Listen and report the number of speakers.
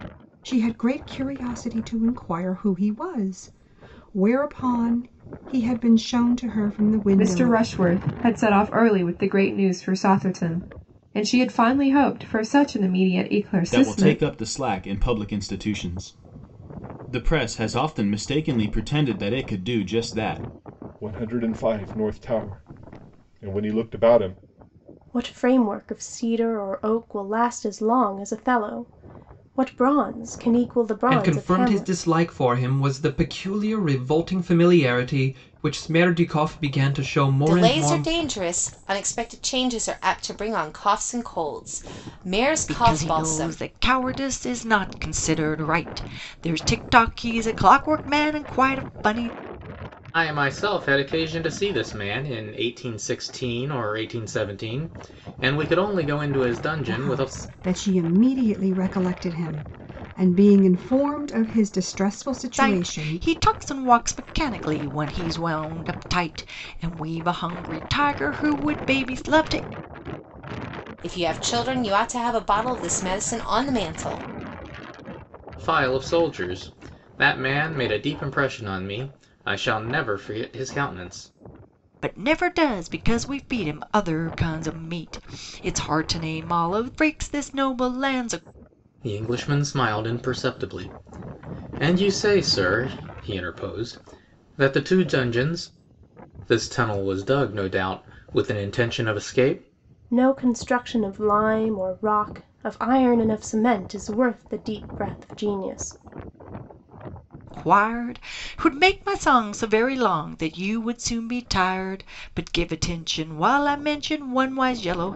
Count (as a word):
nine